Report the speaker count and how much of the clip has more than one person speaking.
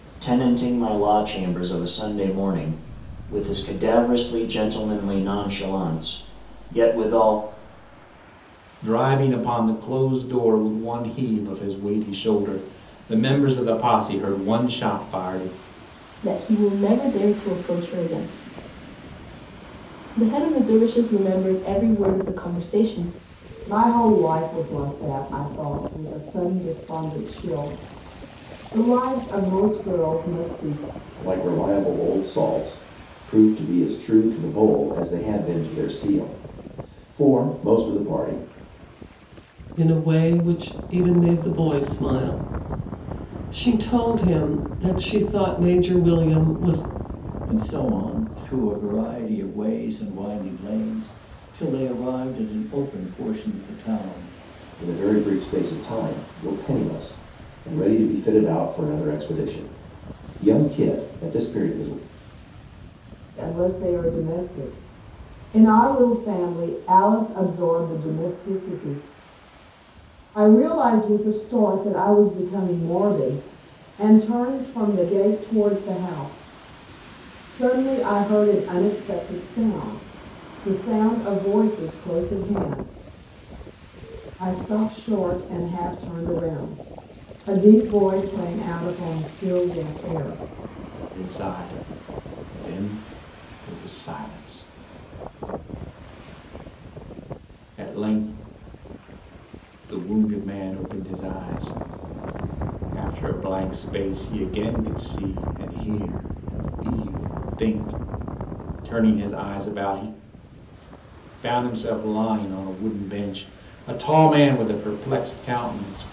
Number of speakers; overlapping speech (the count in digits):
7, no overlap